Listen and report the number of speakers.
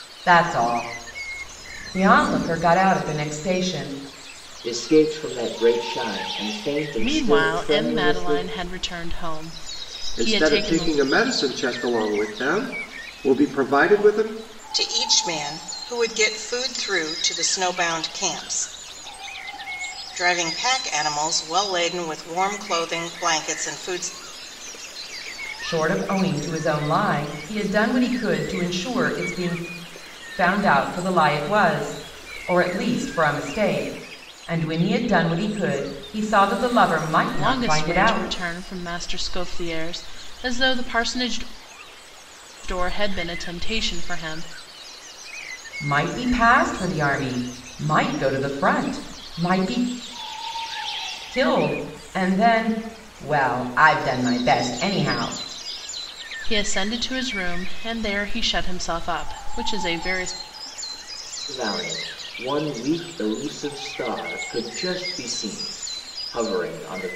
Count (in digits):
5